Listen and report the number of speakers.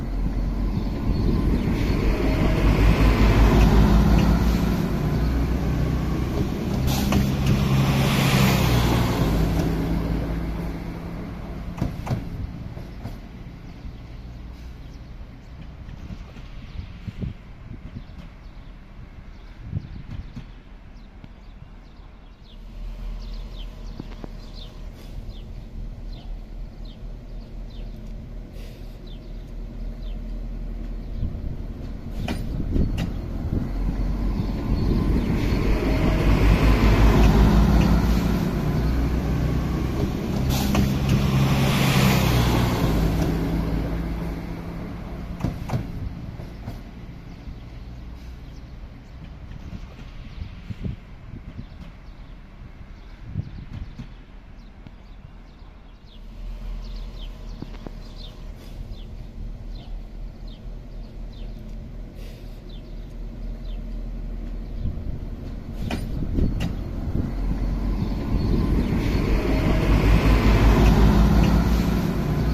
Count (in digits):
0